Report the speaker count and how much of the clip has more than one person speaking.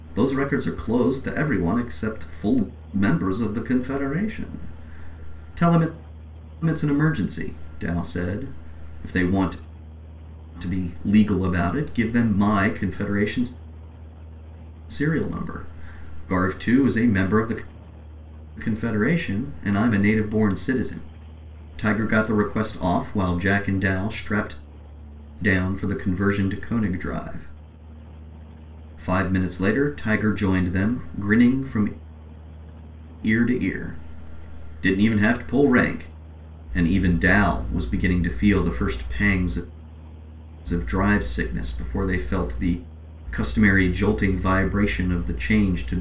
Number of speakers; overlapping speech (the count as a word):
one, no overlap